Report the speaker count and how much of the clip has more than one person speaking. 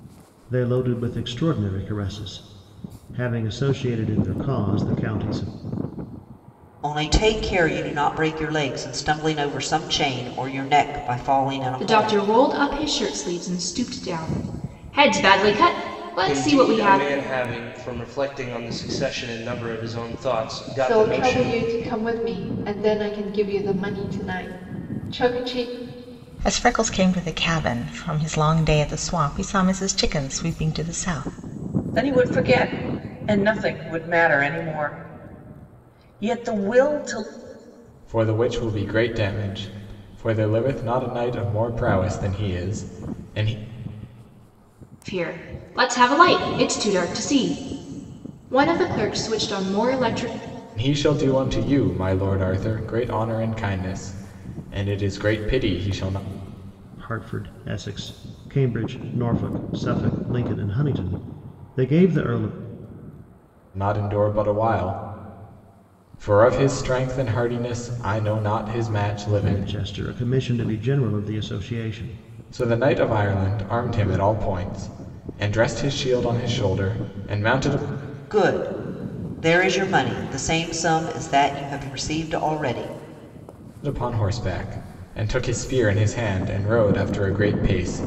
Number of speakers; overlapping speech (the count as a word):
eight, about 3%